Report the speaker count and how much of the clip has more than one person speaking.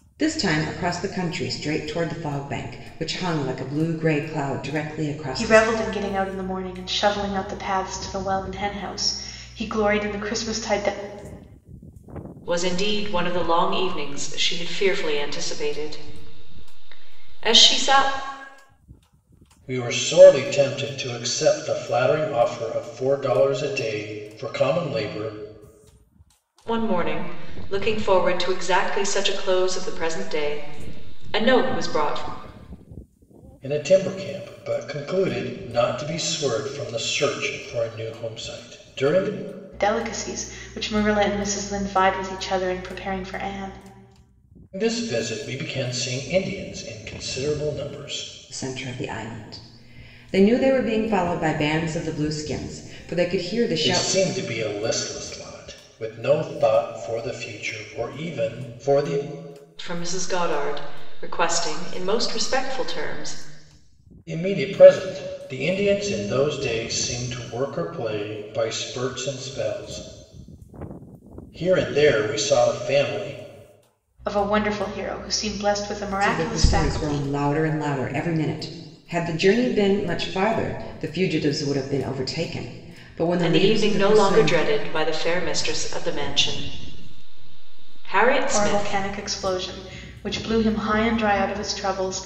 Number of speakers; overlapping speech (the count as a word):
four, about 4%